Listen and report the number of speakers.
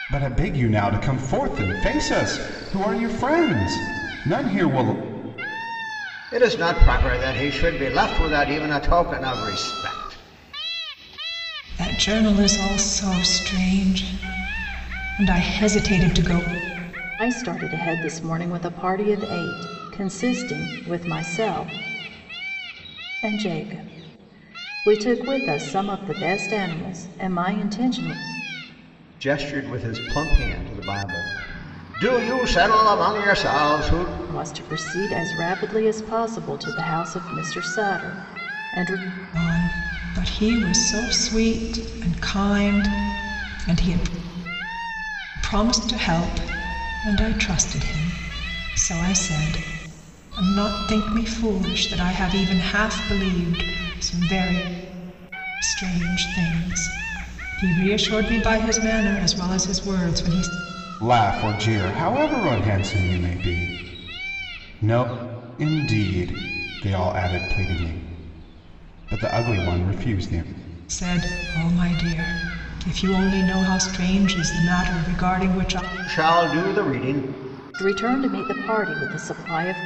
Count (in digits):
4